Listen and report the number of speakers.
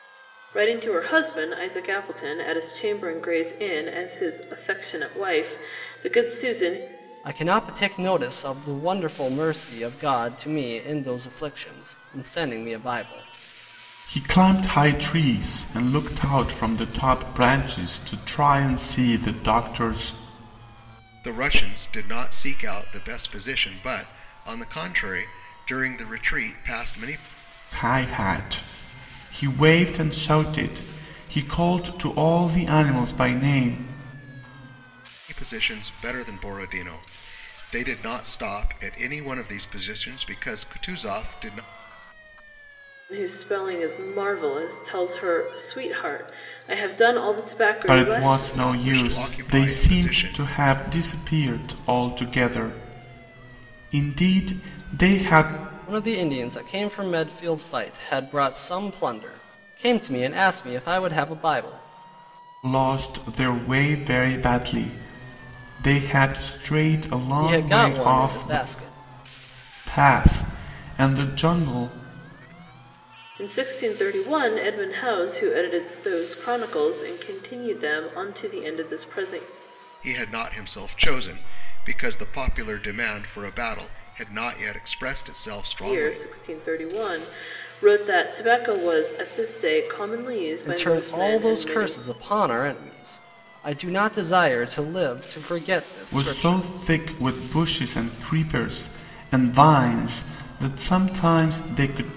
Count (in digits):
4